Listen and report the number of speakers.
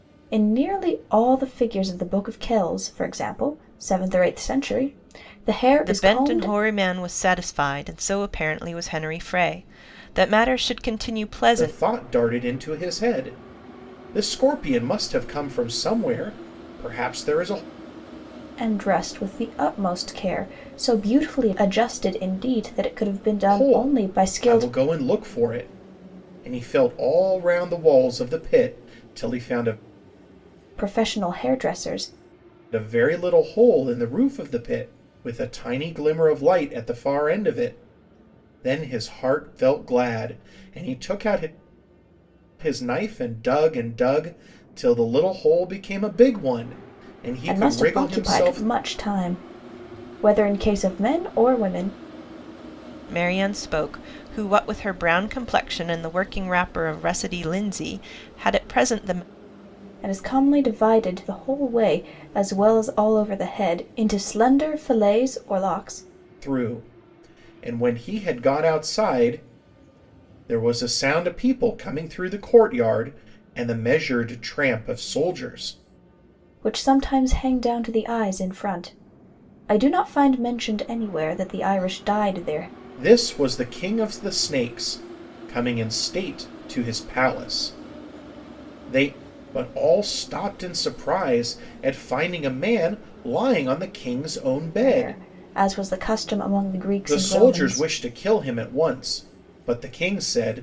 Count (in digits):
3